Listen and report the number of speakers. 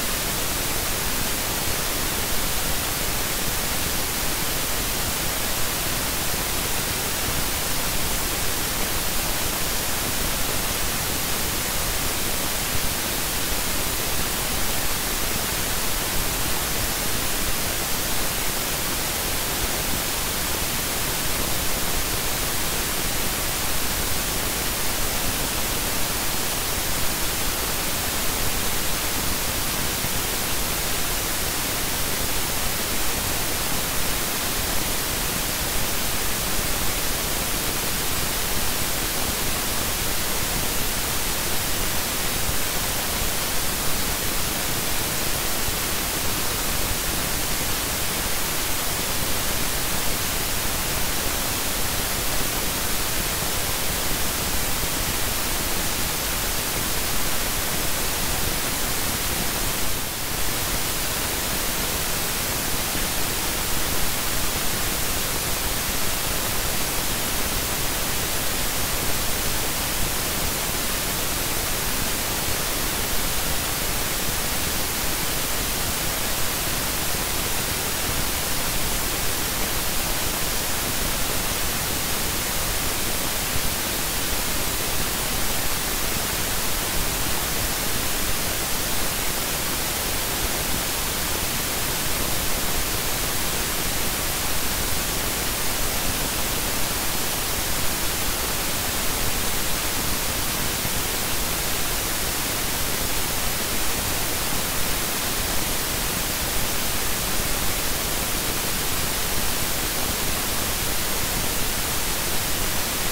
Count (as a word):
zero